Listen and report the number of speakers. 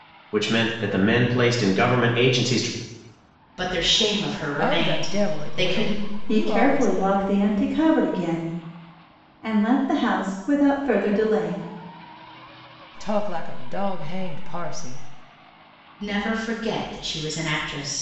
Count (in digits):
4